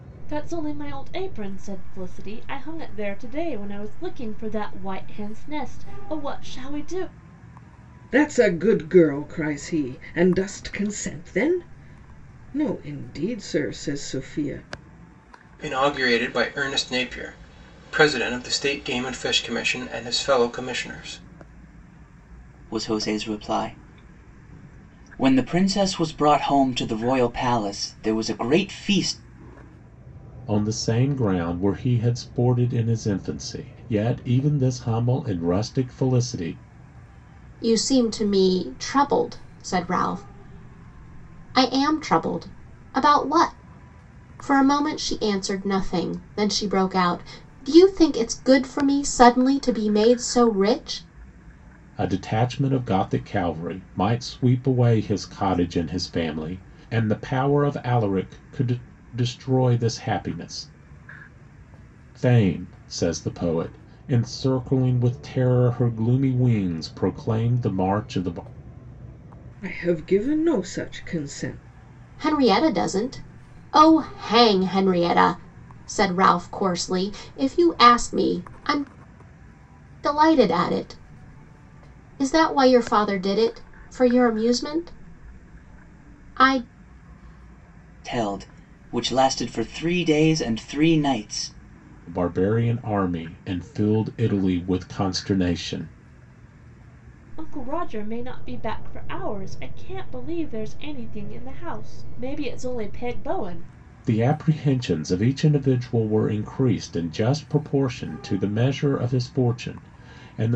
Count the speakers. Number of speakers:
six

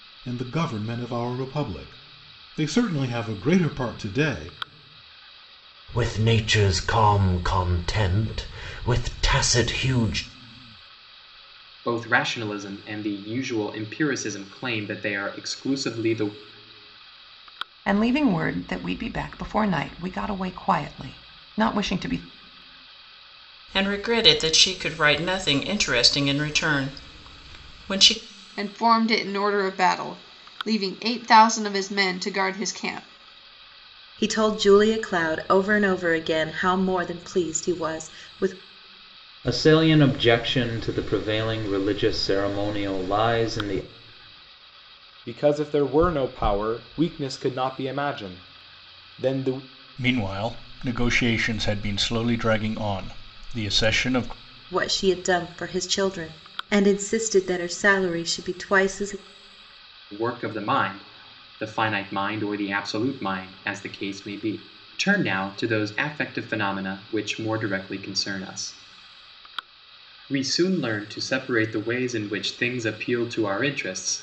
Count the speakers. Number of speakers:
ten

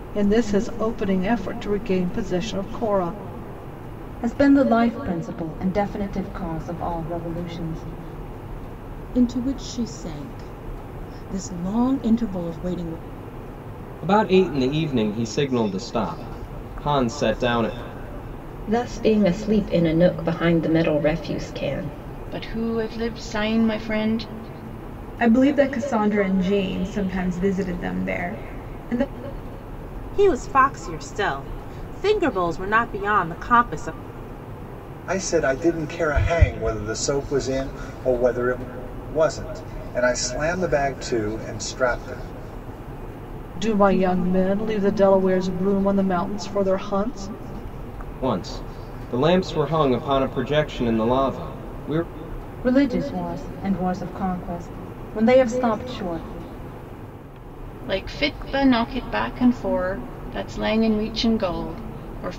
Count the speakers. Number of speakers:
nine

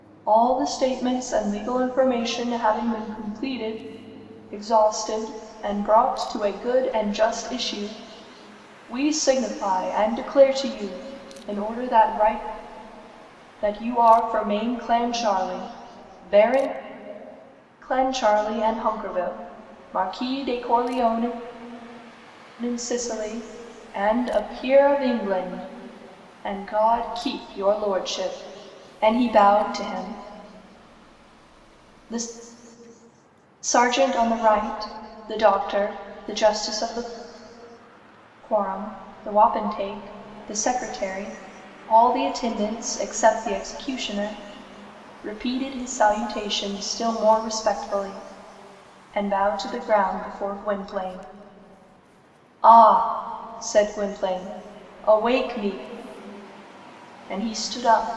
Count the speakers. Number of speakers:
one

